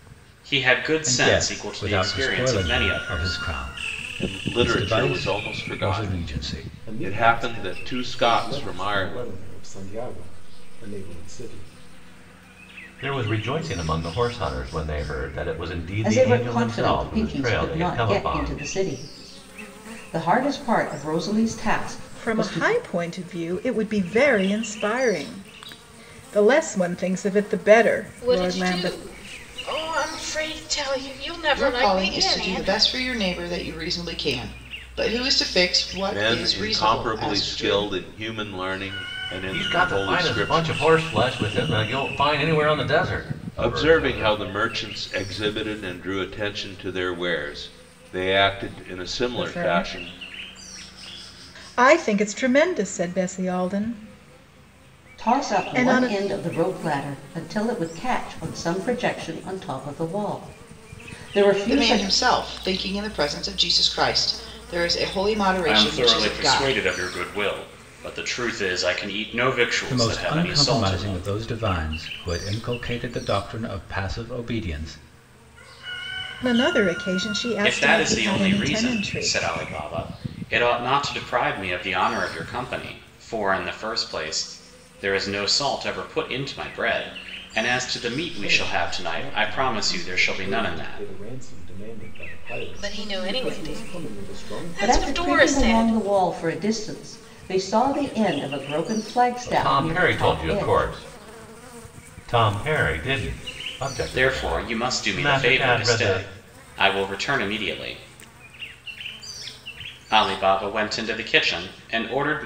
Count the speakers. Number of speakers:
9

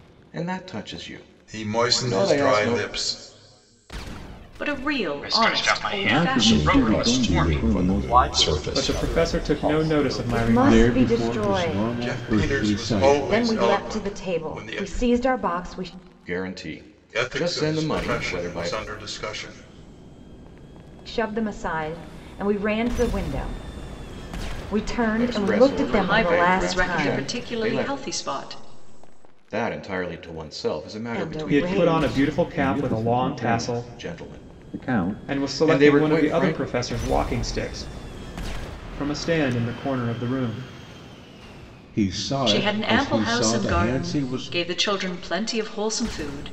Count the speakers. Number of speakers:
10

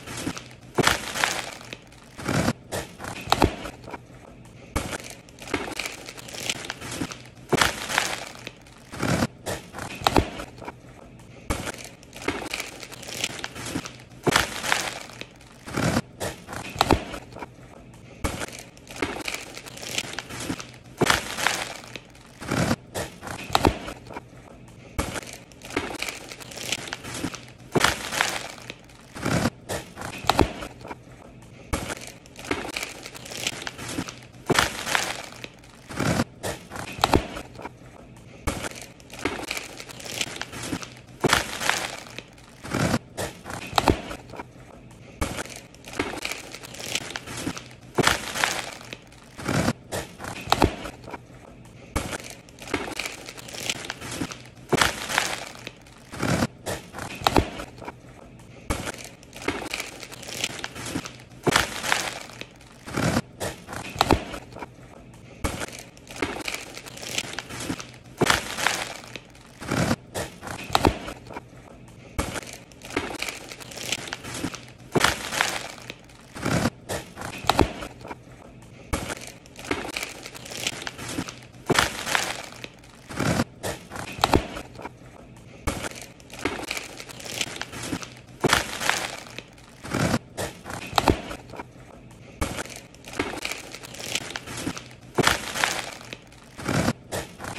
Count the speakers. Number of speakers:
0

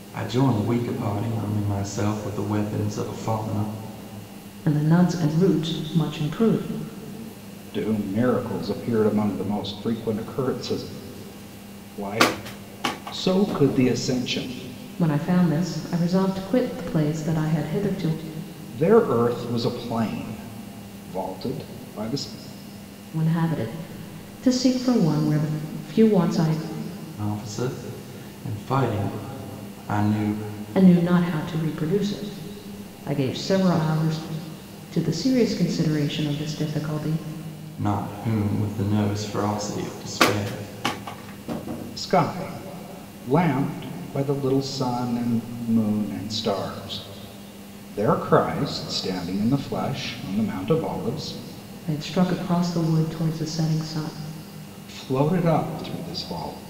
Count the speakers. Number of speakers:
3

